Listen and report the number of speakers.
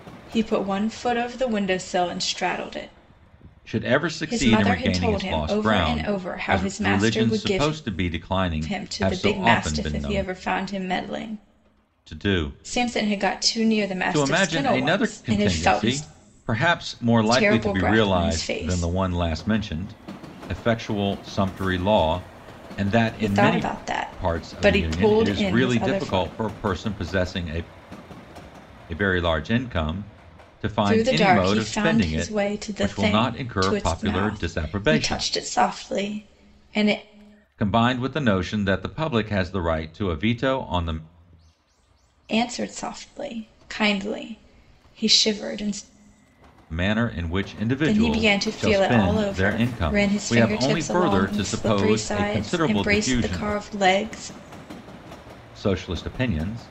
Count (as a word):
two